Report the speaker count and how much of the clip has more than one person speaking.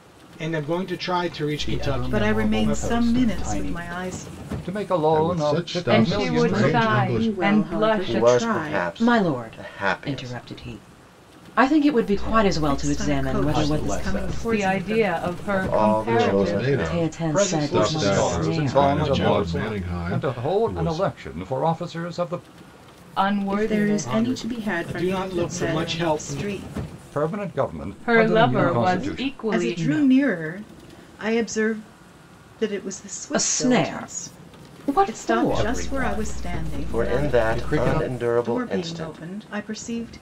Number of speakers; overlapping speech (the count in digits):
9, about 65%